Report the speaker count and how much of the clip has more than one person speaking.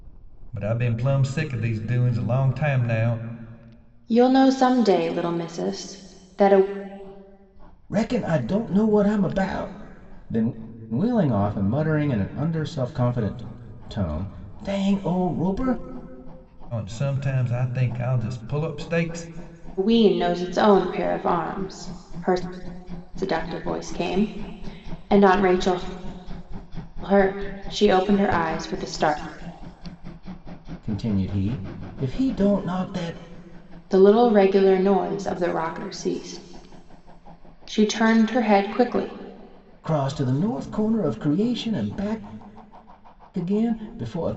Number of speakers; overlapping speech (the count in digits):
3, no overlap